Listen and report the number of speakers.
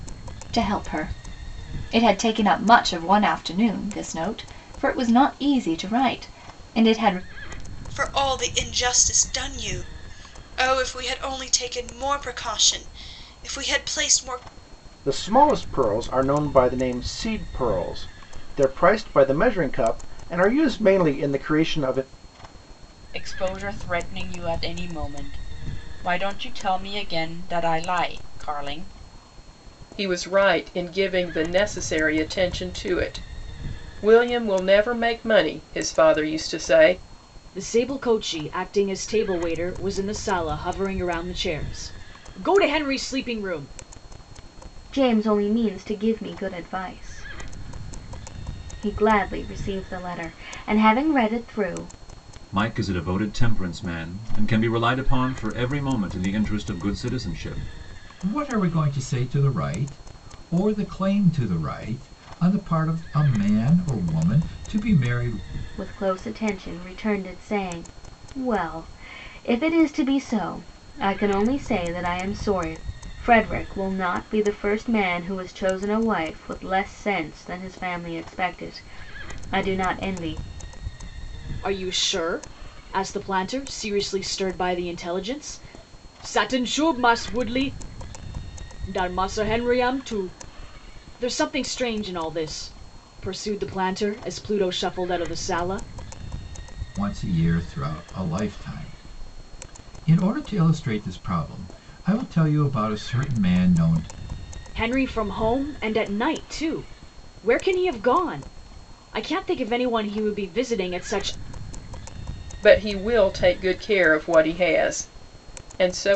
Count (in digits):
9